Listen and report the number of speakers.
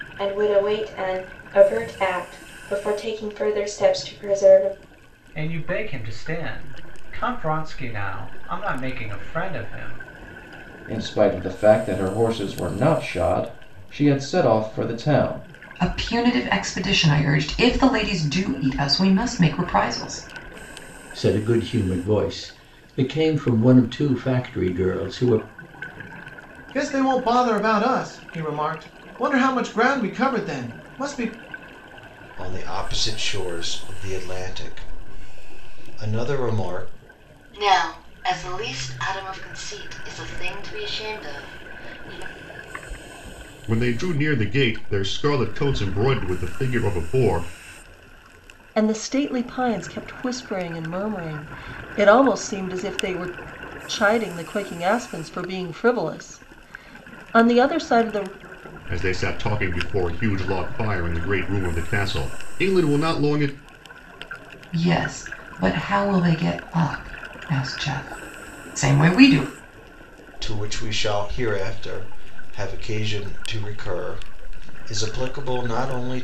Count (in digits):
10